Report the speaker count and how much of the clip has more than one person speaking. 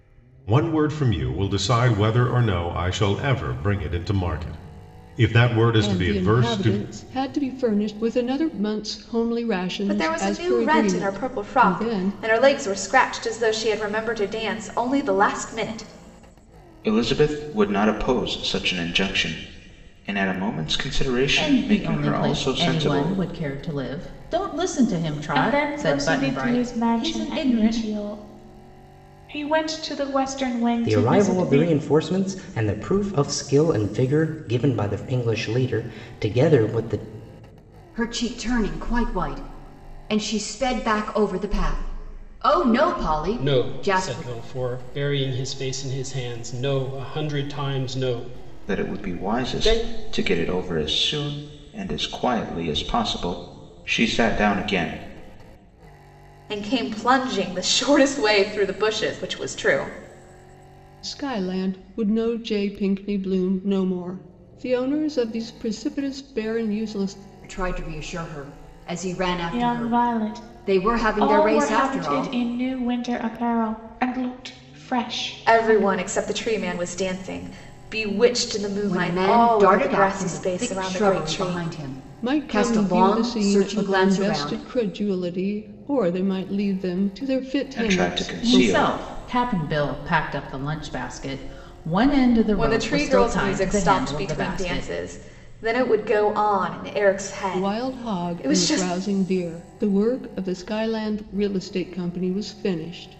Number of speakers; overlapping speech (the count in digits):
9, about 24%